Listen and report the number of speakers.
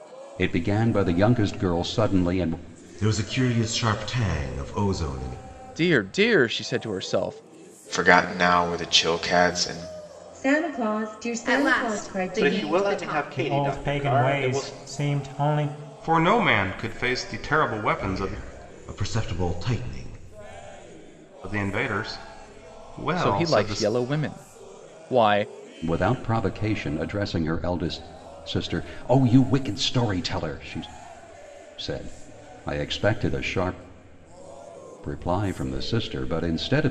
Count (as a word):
nine